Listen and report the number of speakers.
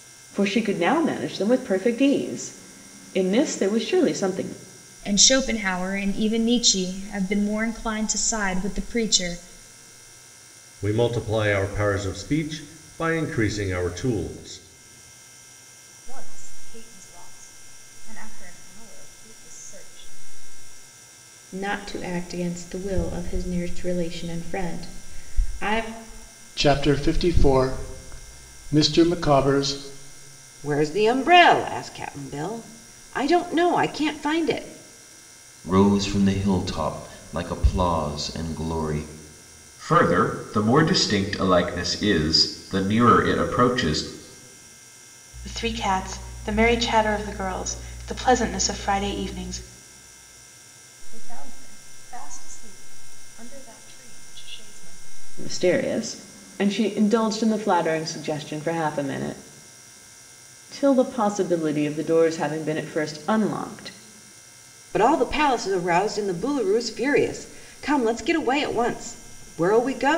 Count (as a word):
ten